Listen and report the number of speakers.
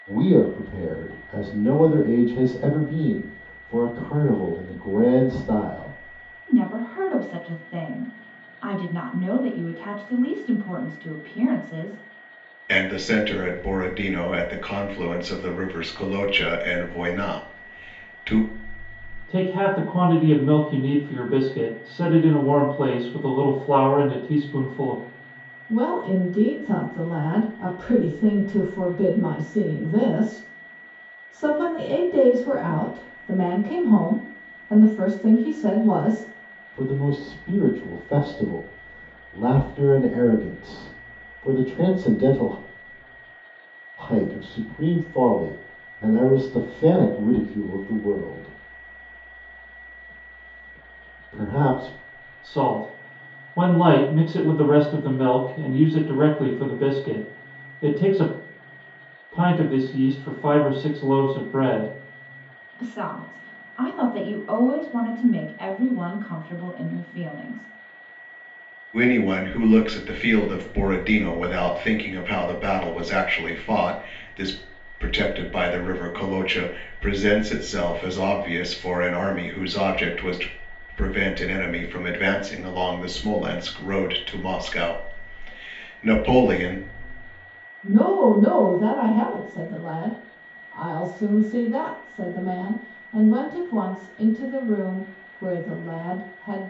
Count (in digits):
5